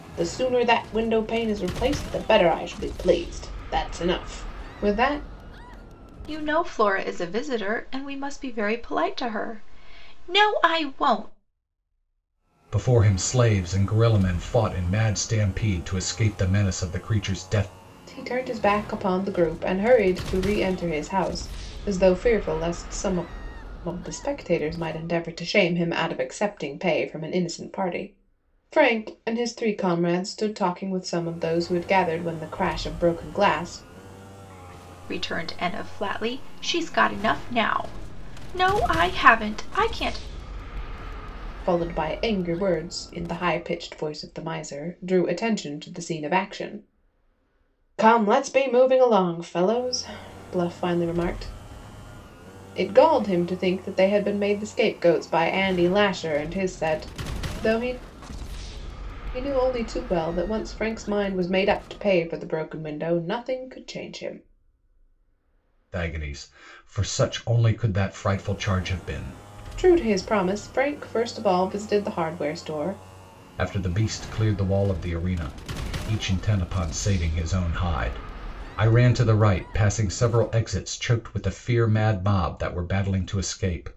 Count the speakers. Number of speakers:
three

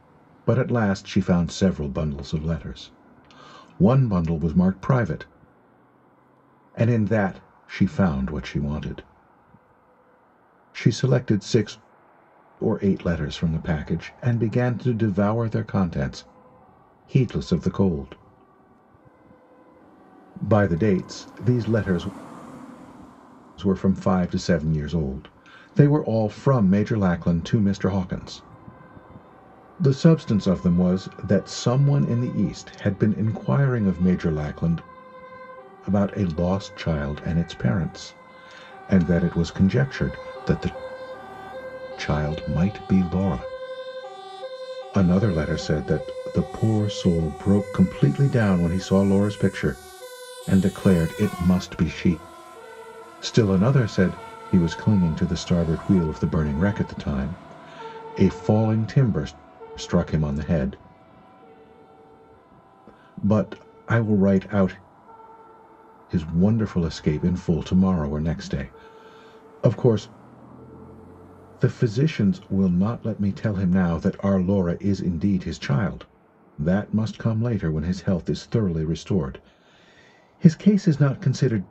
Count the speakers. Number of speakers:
one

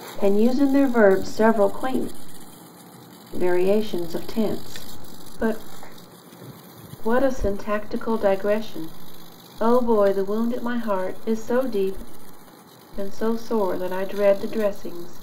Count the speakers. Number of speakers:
one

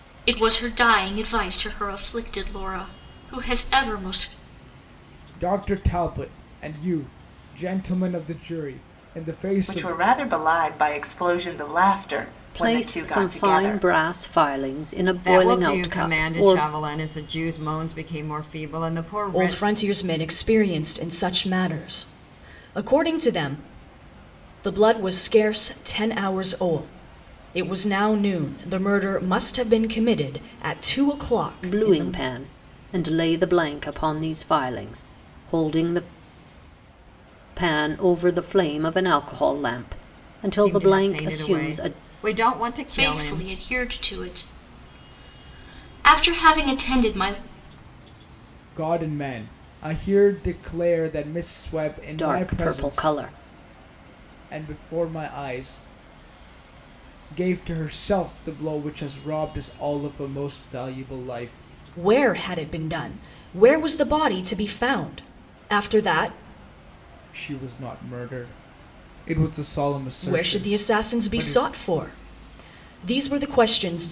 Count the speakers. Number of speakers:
six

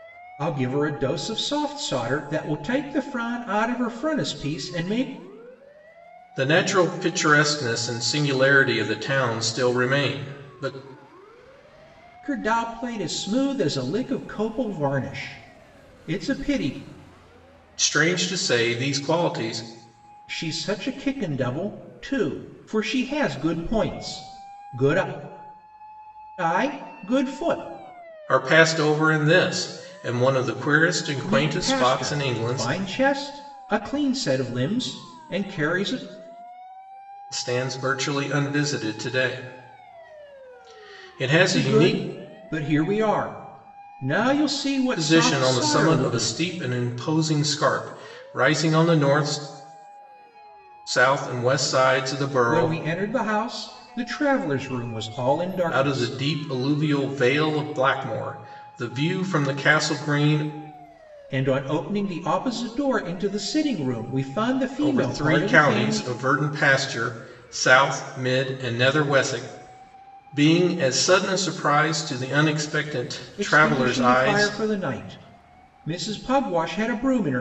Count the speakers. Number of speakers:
two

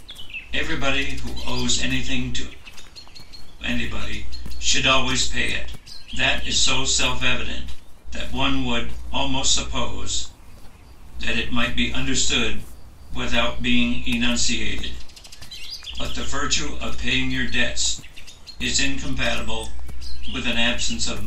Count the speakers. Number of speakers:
one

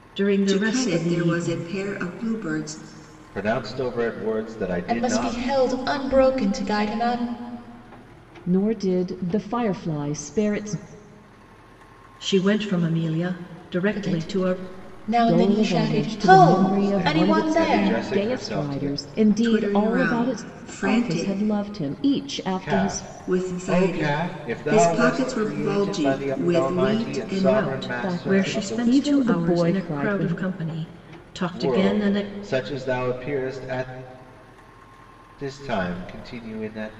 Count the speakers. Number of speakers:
five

